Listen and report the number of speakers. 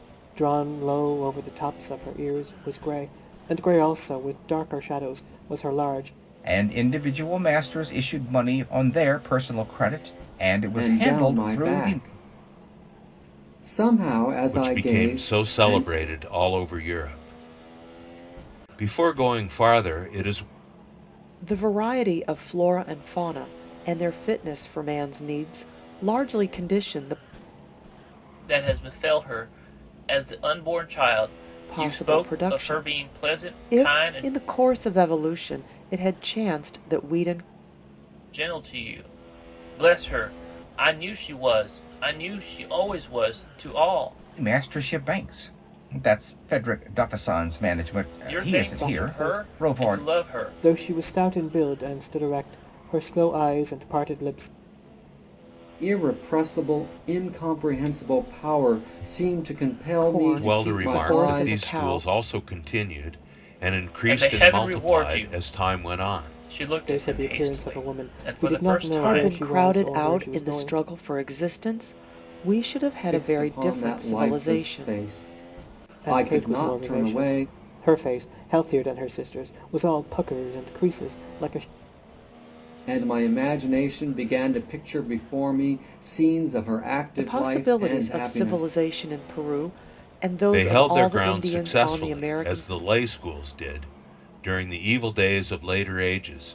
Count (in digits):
6